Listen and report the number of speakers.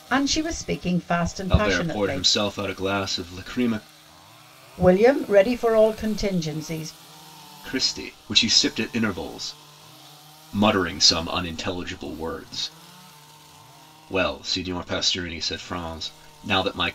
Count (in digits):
2